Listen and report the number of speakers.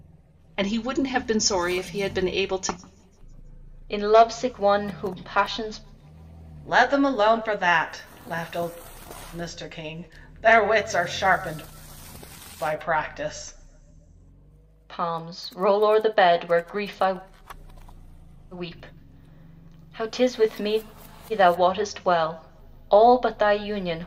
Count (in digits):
3